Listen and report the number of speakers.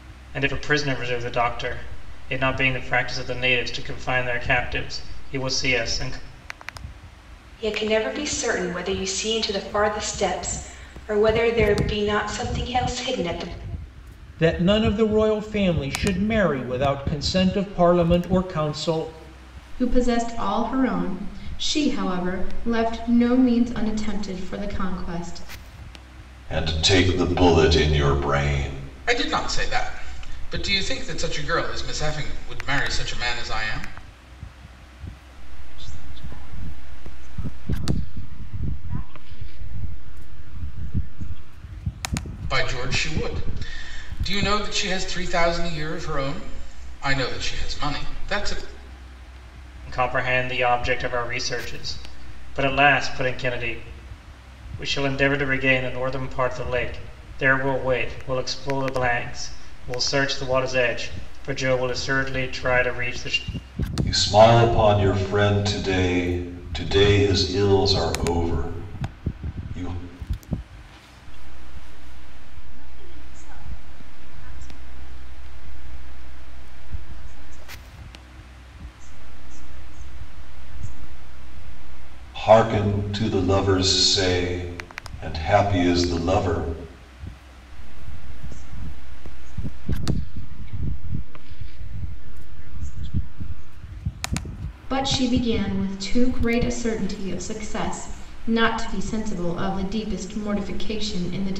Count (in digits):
7